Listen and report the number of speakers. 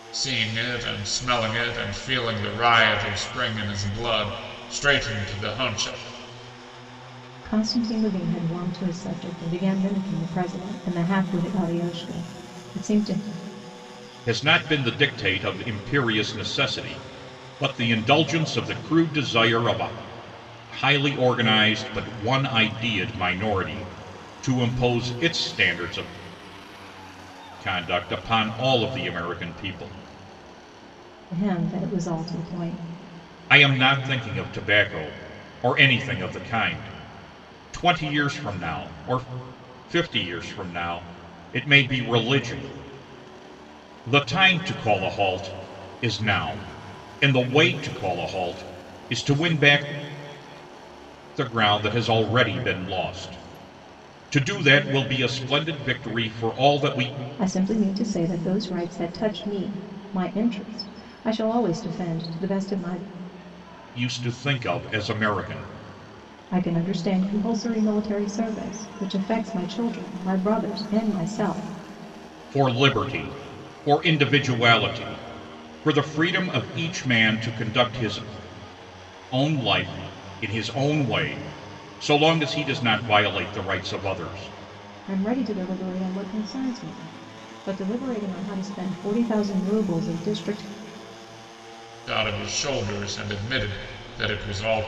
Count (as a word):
three